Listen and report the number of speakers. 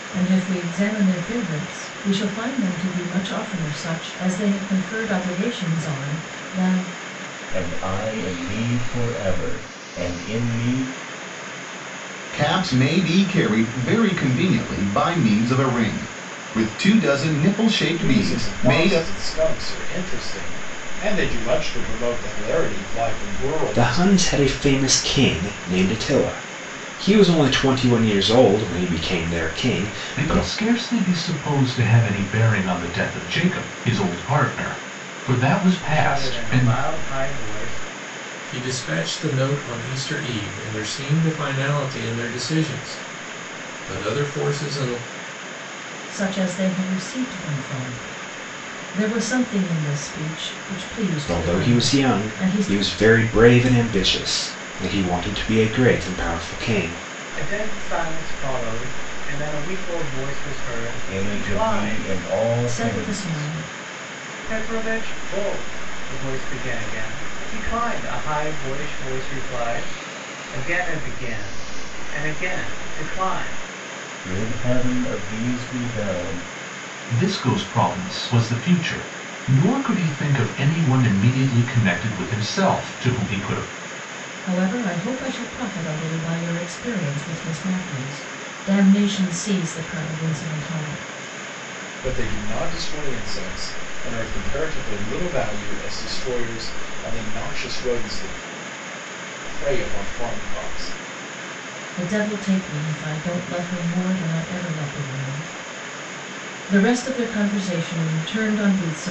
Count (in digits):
8